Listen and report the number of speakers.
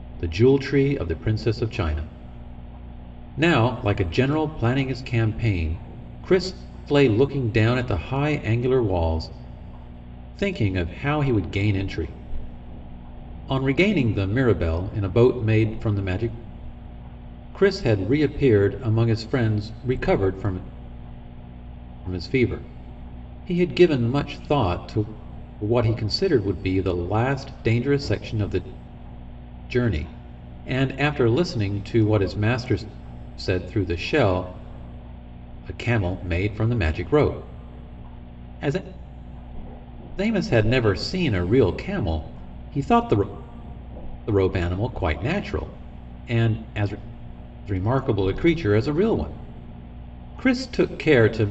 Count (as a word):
one